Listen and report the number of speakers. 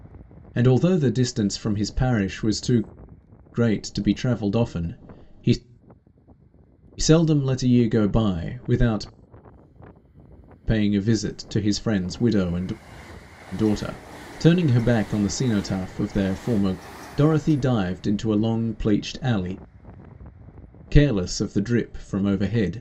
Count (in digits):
1